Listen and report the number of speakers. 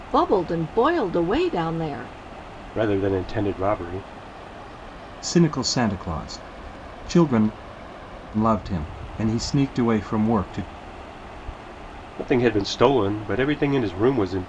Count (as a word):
three